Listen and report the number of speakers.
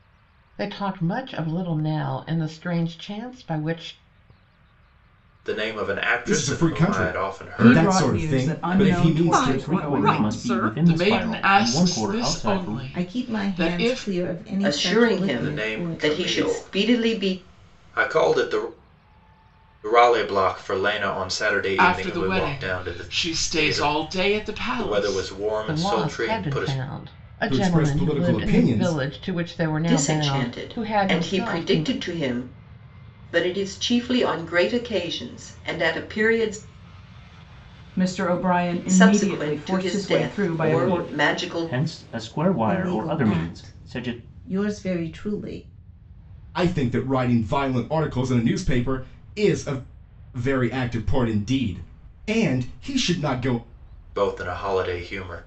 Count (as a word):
nine